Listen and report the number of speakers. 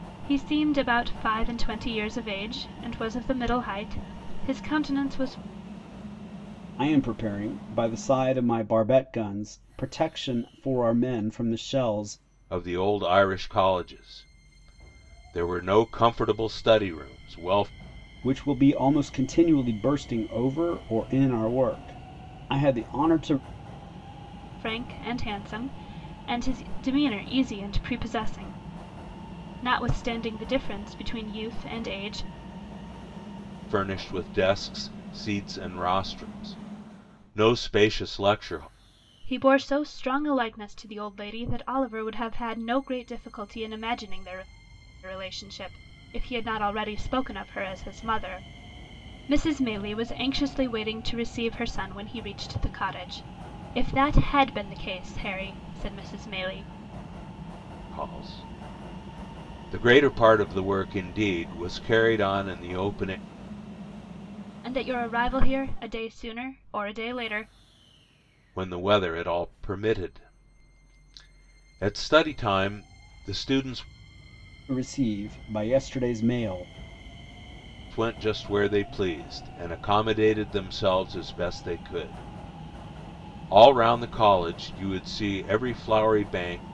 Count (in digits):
3